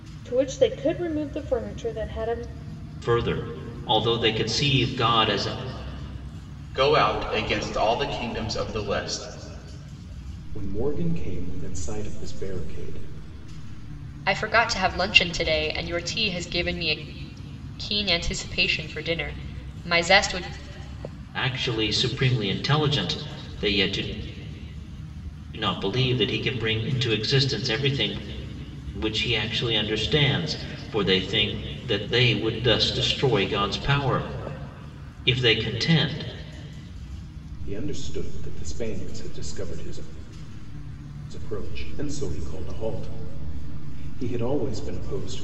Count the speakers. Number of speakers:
five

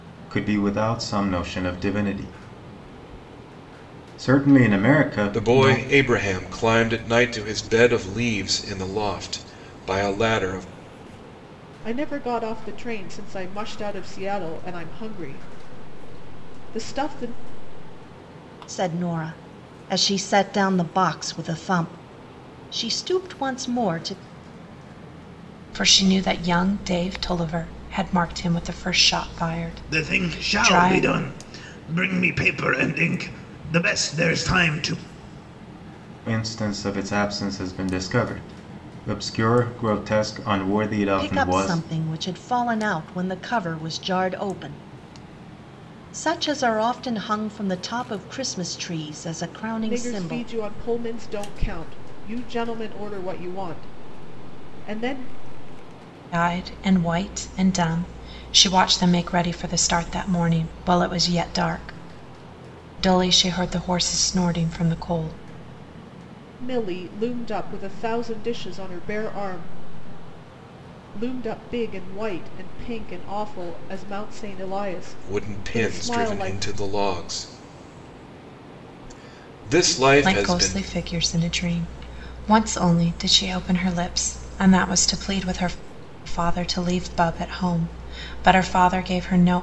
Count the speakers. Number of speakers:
six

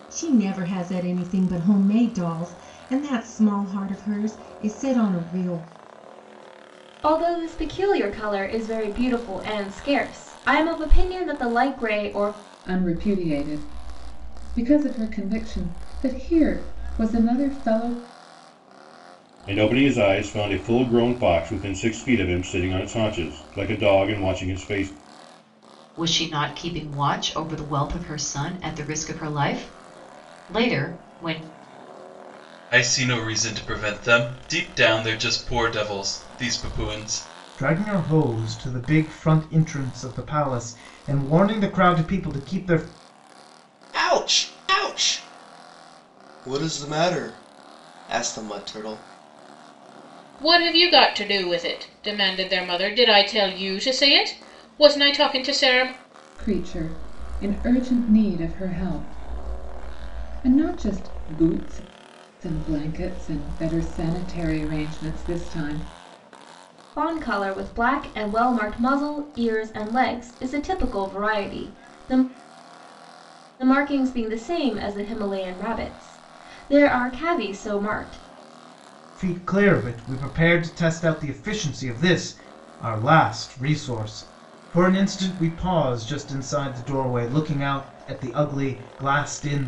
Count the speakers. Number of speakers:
nine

